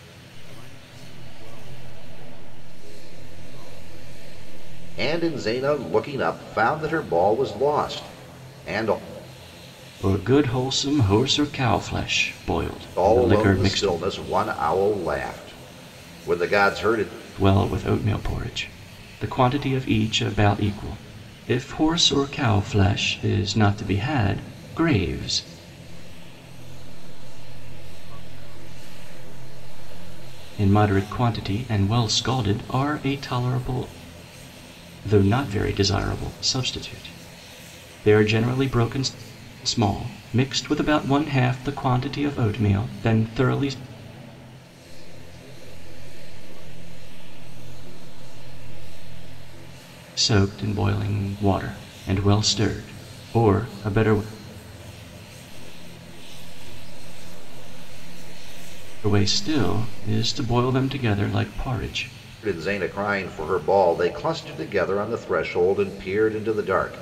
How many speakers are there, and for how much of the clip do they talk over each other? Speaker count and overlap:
3, about 2%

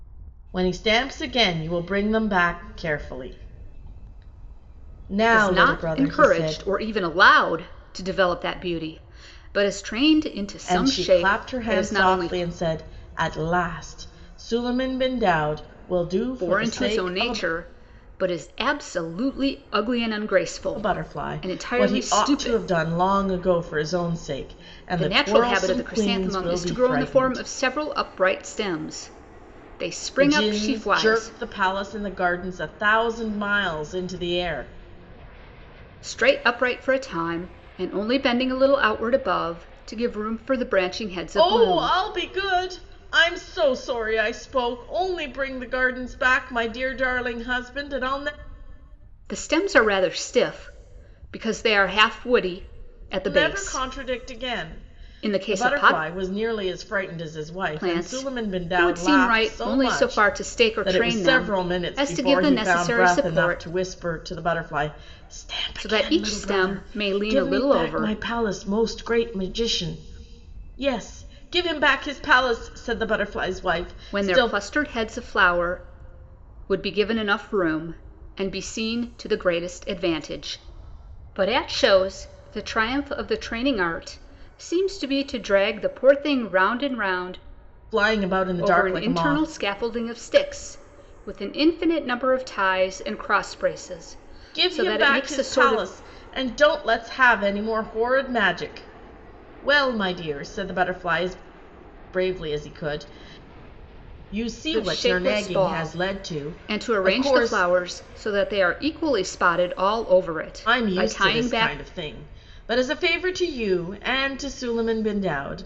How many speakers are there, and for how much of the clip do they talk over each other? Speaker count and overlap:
2, about 24%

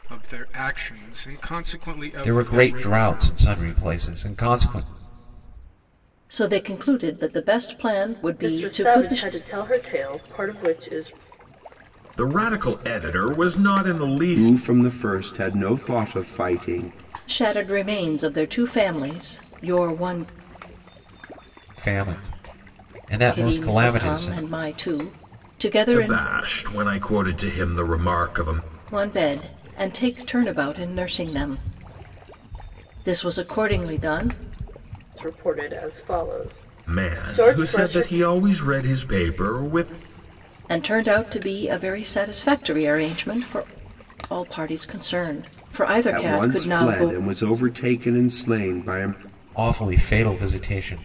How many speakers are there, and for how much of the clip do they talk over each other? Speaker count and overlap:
6, about 11%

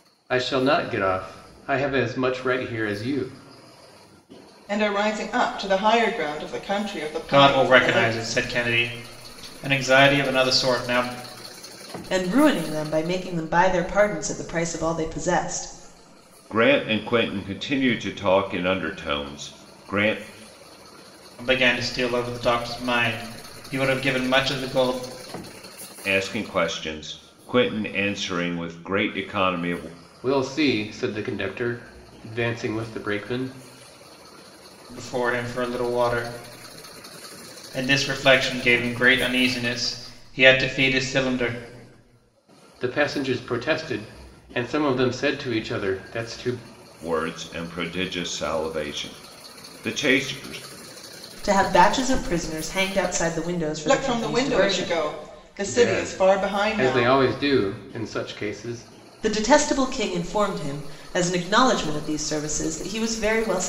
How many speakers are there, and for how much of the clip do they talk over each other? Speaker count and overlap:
5, about 6%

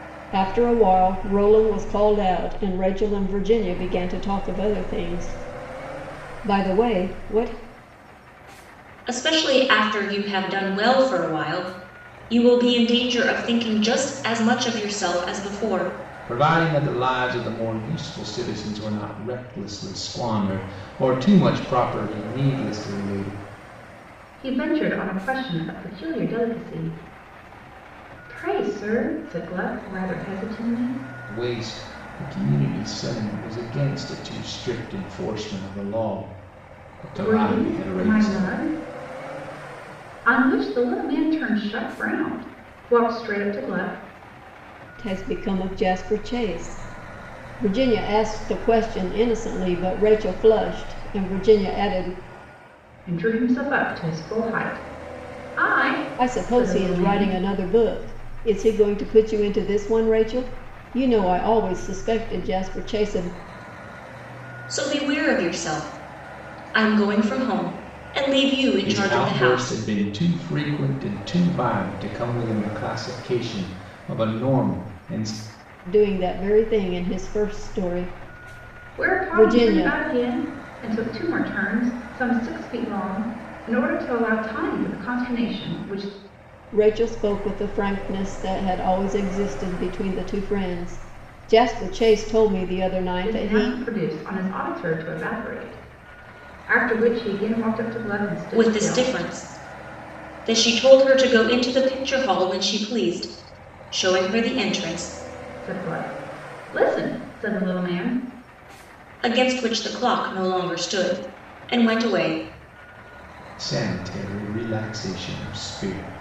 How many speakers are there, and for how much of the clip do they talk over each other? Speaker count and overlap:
4, about 5%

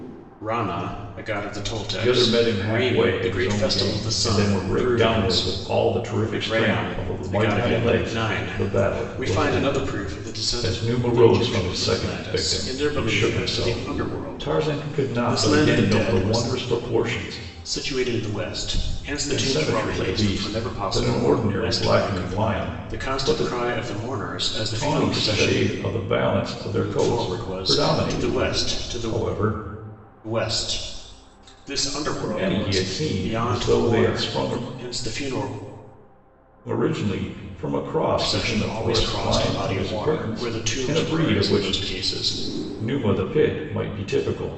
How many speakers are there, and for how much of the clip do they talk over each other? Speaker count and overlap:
2, about 60%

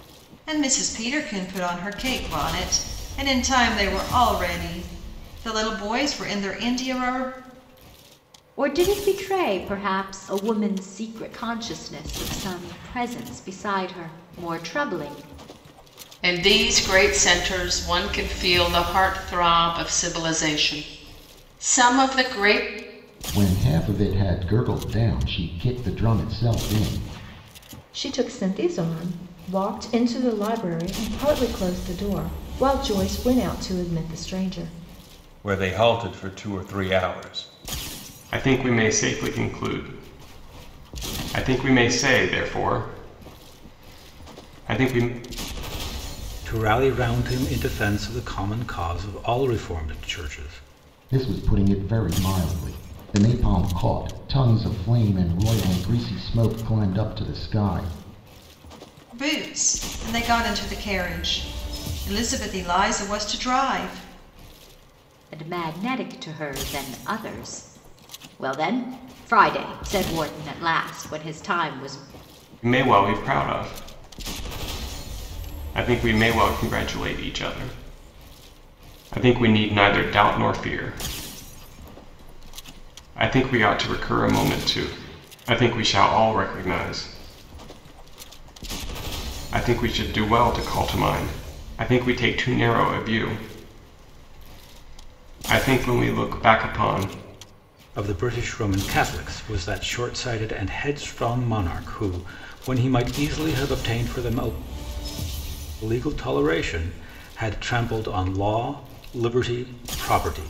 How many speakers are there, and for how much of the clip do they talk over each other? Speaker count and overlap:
8, no overlap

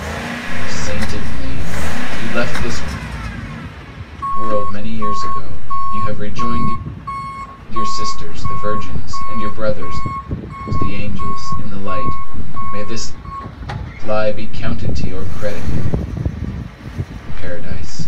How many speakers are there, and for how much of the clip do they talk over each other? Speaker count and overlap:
1, no overlap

